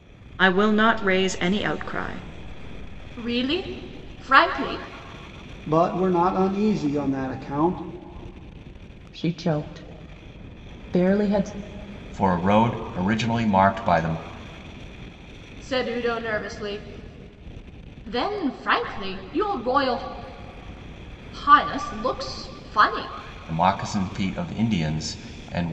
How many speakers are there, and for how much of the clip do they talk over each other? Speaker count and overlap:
5, no overlap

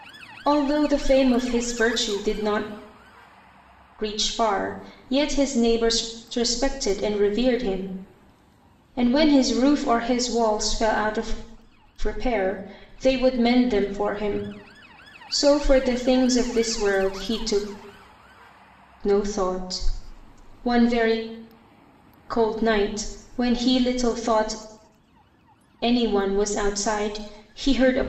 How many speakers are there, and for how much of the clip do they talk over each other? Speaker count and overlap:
1, no overlap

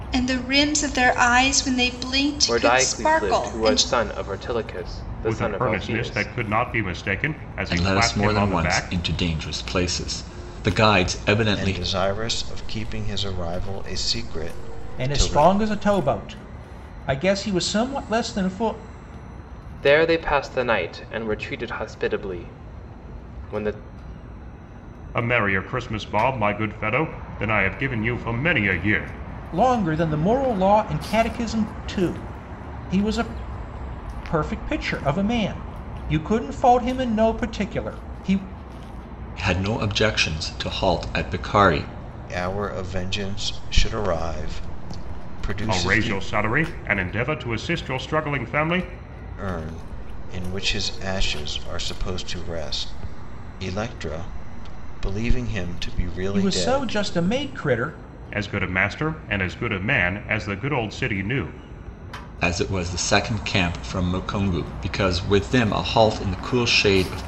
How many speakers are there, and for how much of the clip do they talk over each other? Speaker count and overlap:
6, about 9%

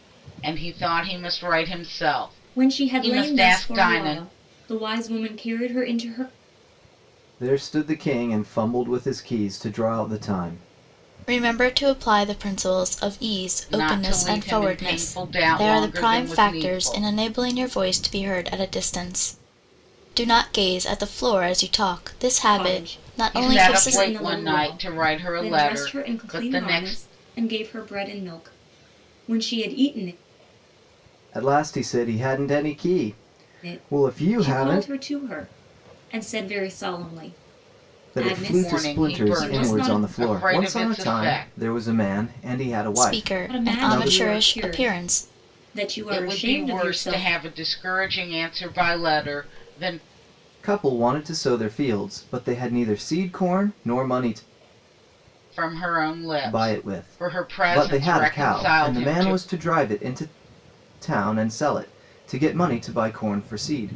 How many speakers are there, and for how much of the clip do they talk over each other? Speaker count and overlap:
4, about 33%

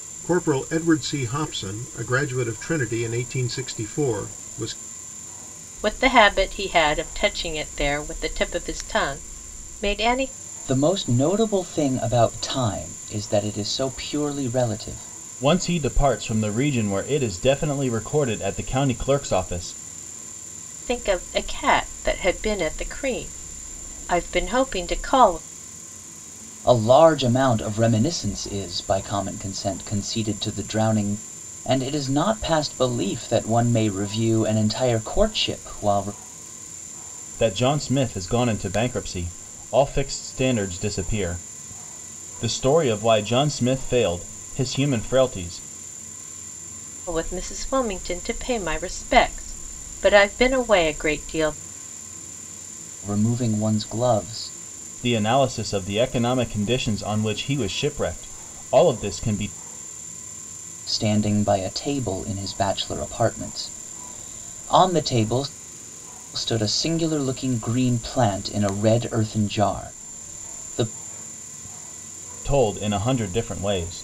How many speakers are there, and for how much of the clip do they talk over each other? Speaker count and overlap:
4, no overlap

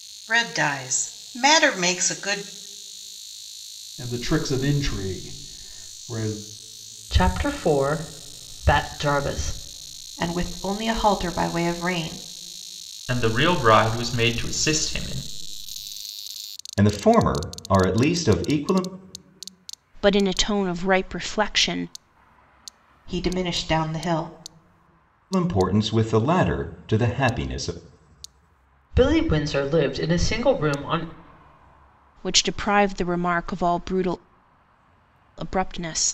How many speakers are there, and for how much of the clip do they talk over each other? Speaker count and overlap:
7, no overlap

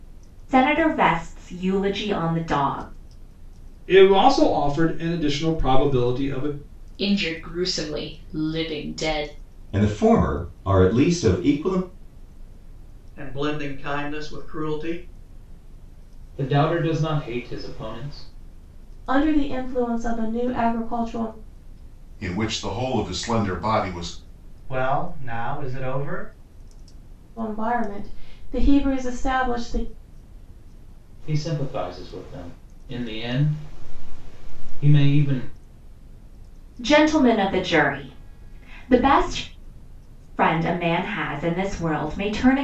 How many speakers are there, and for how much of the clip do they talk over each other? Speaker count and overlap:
9, no overlap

